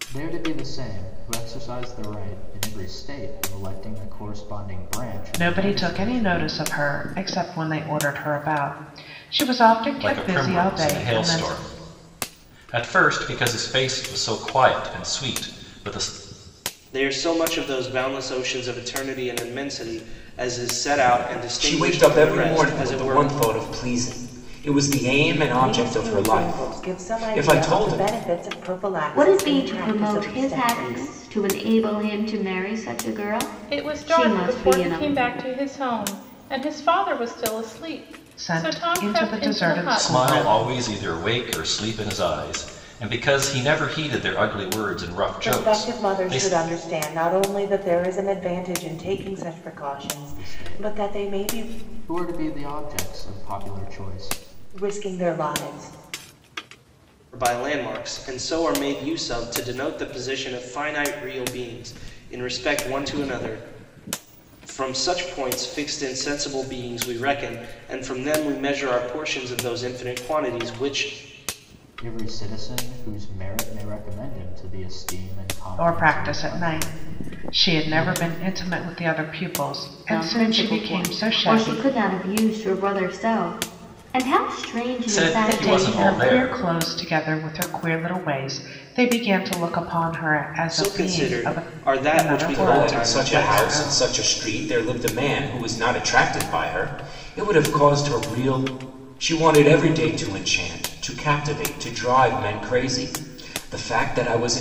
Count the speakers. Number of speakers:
eight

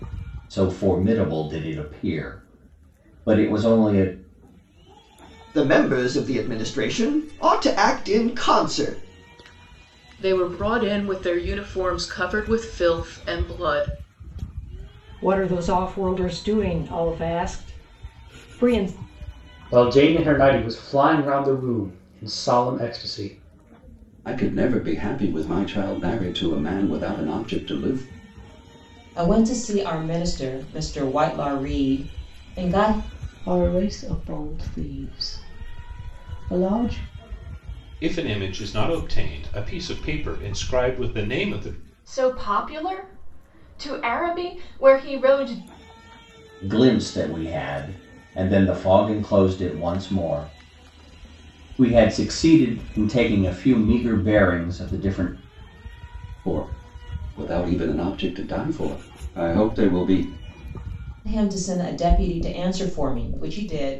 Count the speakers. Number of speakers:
ten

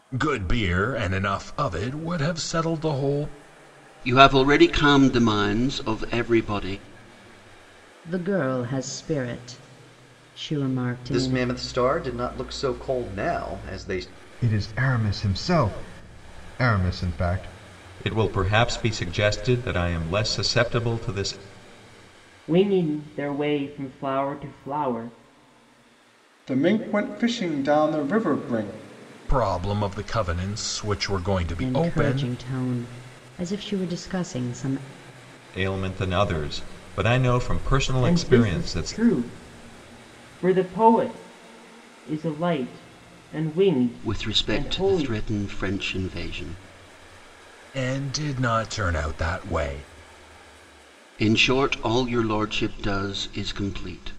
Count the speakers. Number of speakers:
eight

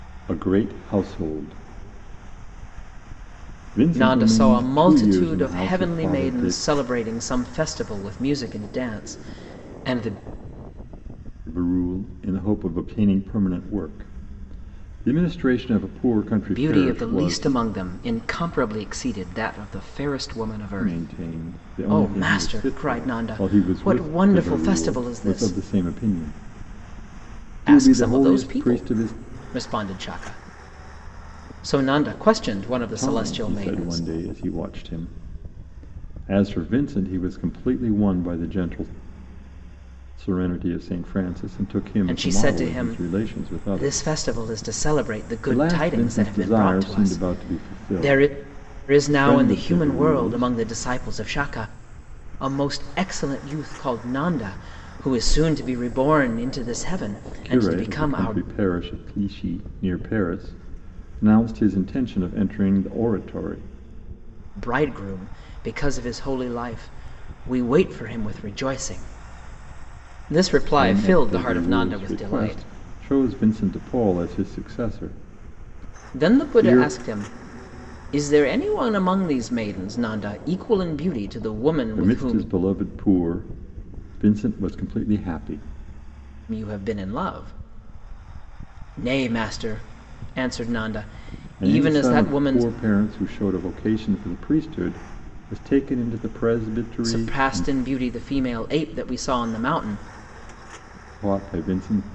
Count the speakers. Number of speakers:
two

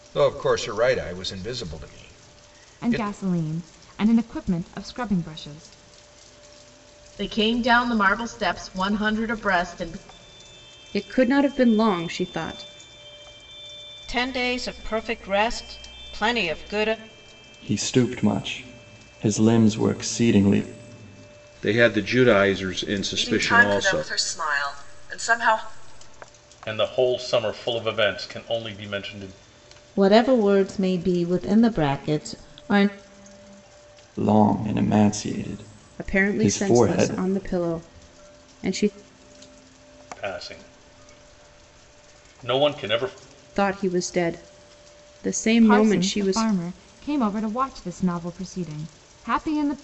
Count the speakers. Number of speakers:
ten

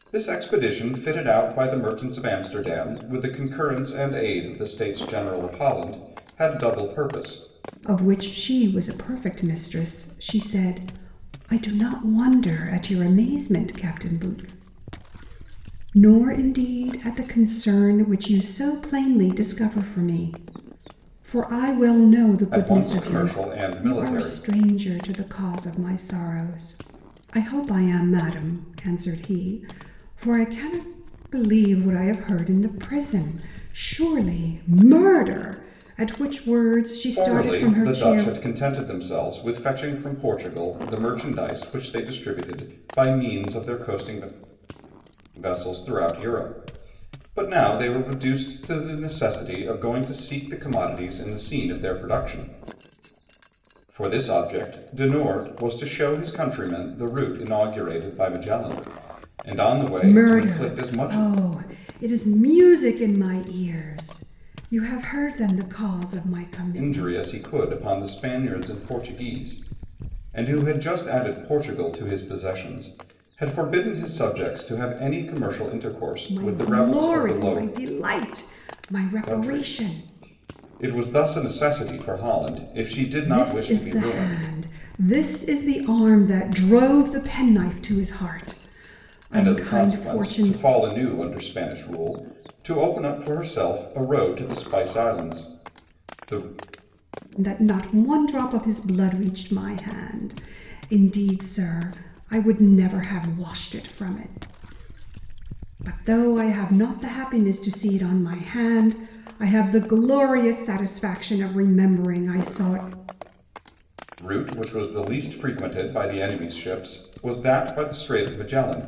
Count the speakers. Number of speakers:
two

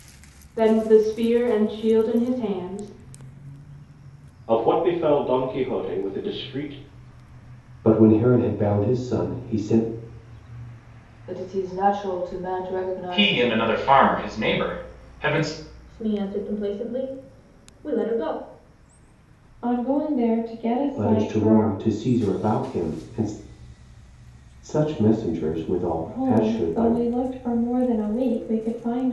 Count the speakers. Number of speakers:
seven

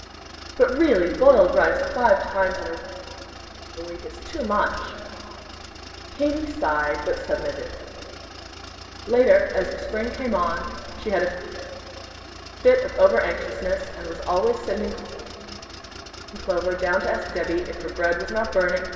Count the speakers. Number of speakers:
one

